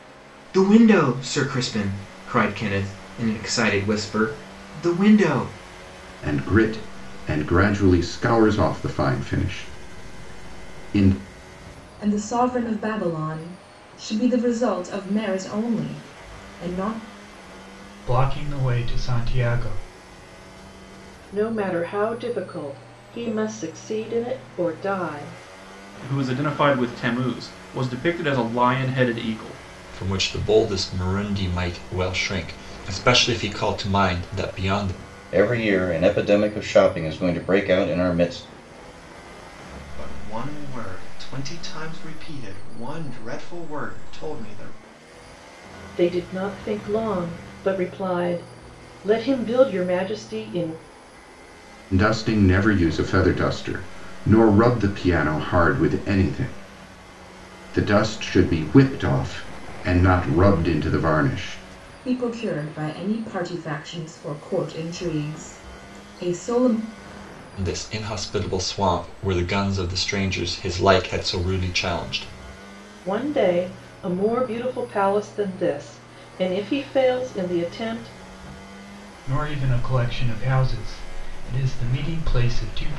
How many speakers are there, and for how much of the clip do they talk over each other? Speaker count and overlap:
nine, no overlap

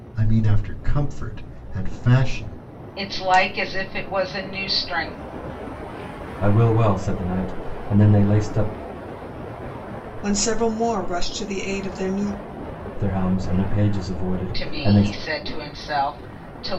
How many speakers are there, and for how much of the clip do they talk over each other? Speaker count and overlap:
four, about 4%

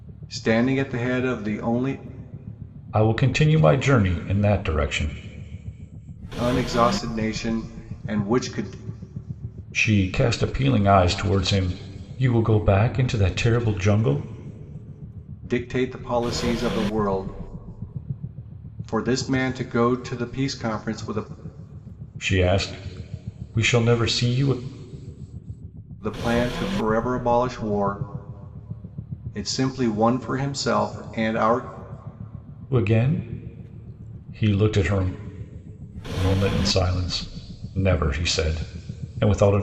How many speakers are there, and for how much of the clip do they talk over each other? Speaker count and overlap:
two, no overlap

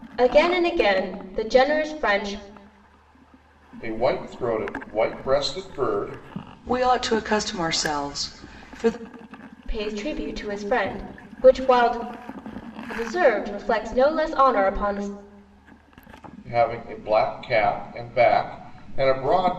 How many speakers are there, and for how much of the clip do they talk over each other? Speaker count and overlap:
three, no overlap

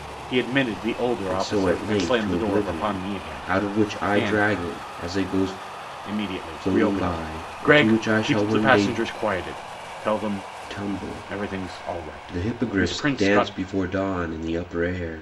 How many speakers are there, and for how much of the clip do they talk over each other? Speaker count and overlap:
two, about 50%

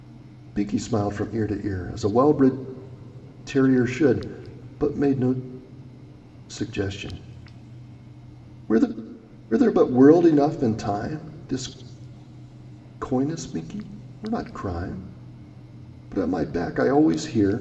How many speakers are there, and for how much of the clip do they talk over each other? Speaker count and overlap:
one, no overlap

